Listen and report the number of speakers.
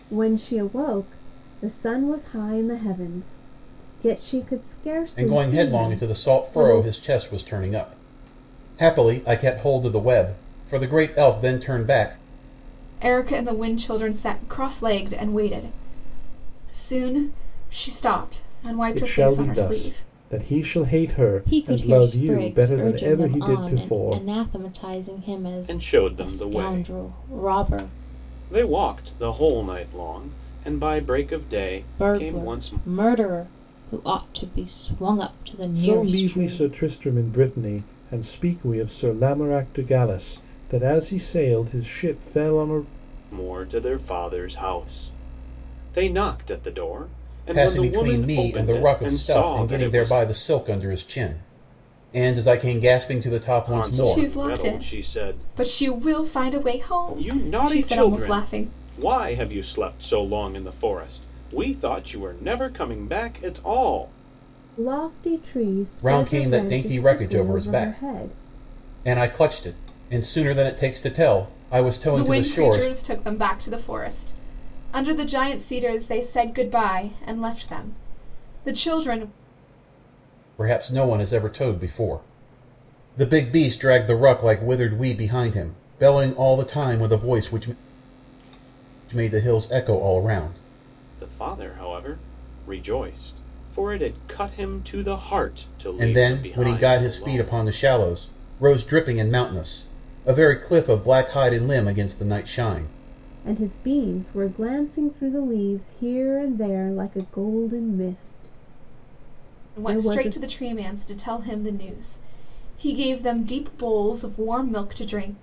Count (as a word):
six